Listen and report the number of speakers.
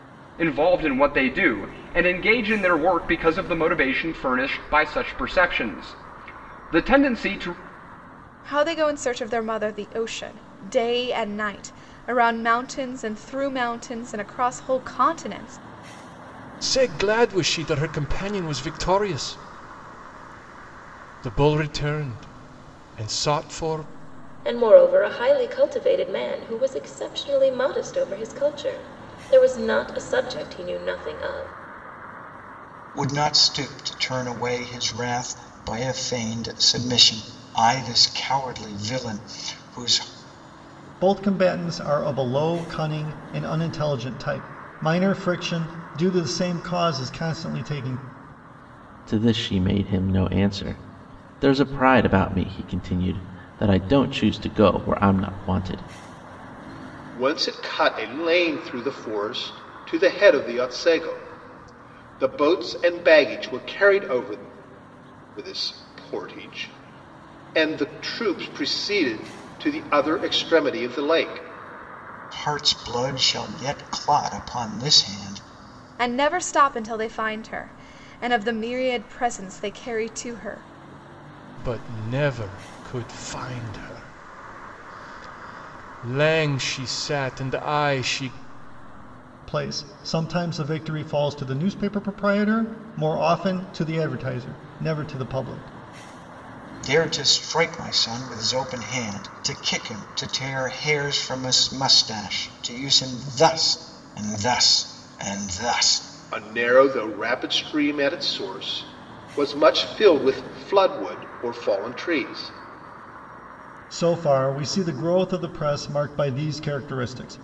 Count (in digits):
8